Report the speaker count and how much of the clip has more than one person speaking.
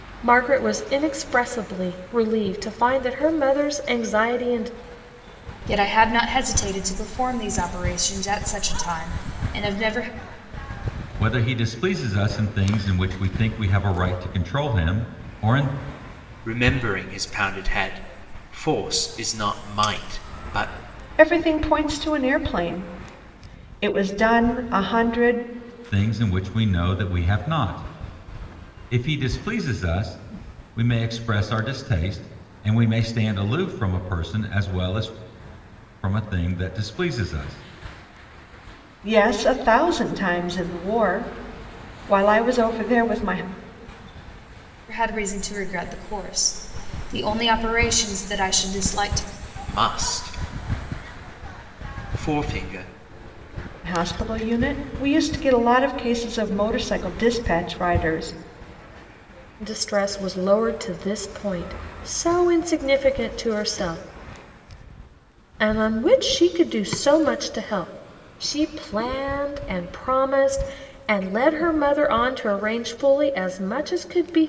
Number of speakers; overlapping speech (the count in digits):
5, no overlap